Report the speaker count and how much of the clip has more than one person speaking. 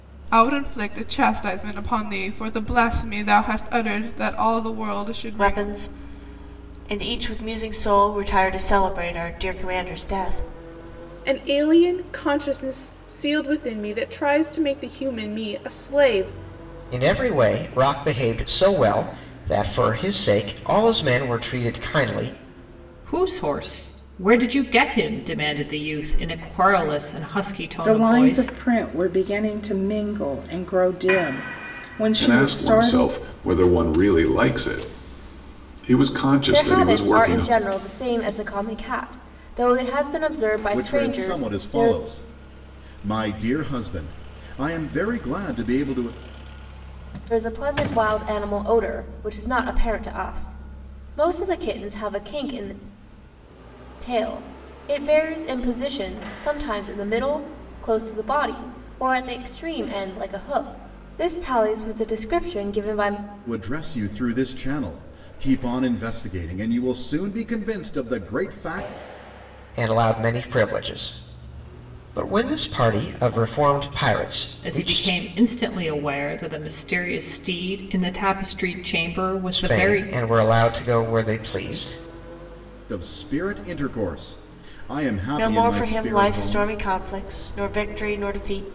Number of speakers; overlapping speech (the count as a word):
nine, about 8%